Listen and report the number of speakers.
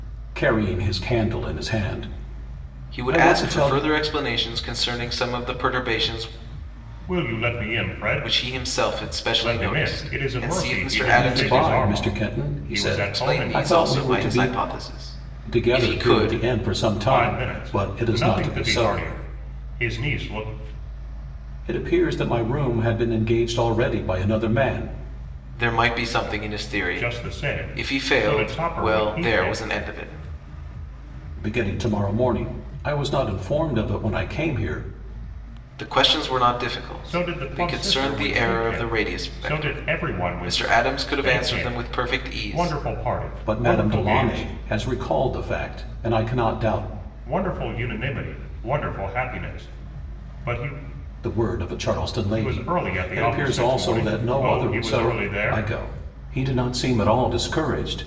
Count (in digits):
3